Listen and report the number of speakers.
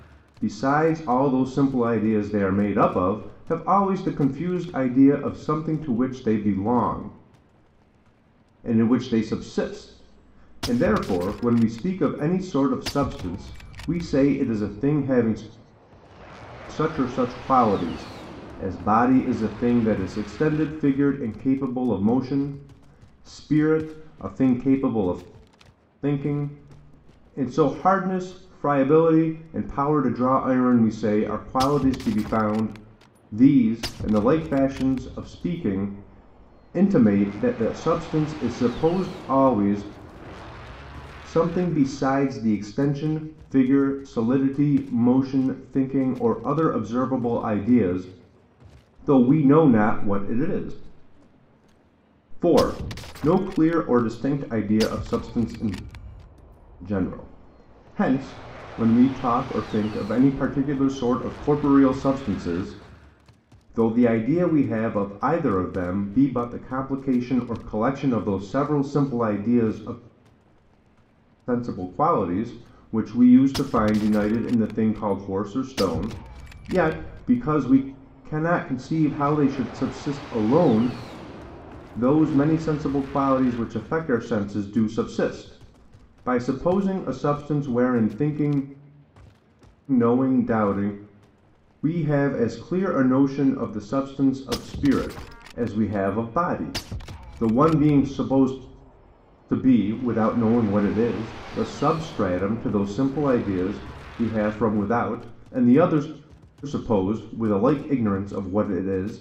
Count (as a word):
one